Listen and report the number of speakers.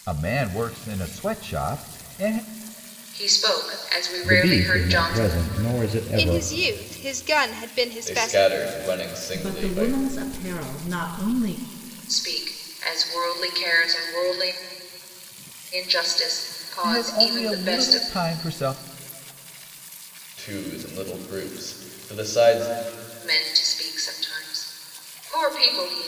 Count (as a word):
six